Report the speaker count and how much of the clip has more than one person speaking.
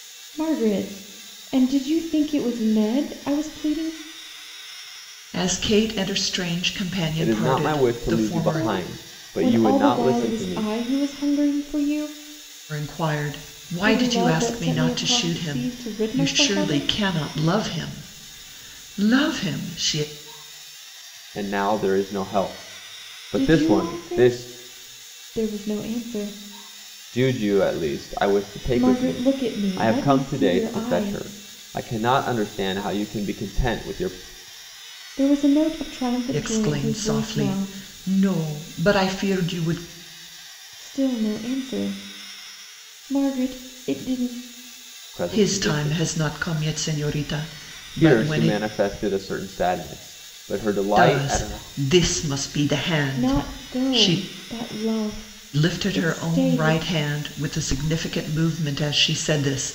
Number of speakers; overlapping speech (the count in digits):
3, about 28%